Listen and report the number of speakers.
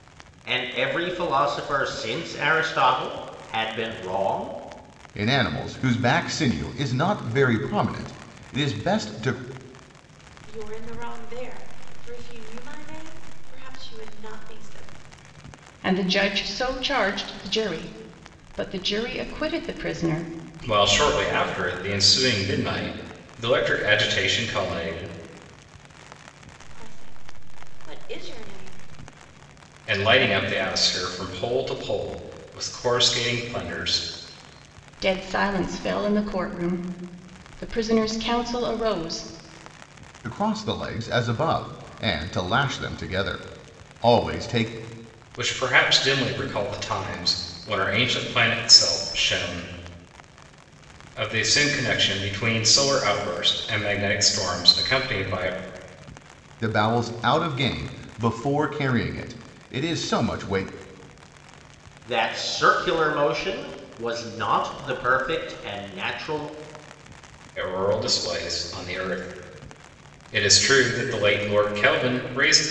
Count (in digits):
5